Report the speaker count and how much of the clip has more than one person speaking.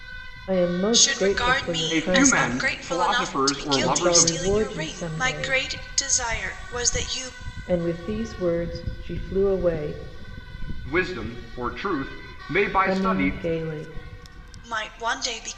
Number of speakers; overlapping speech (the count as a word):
three, about 34%